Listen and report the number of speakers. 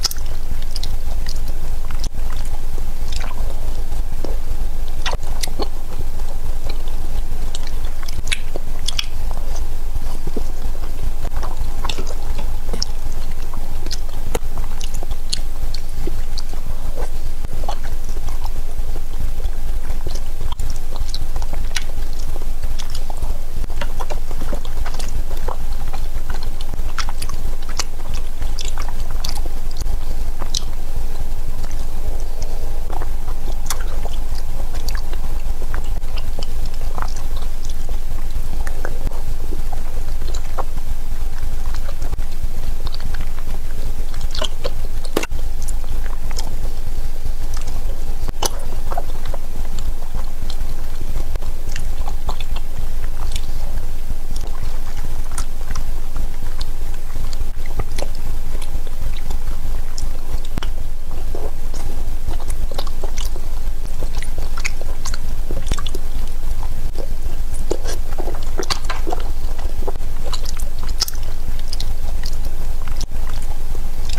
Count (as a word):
zero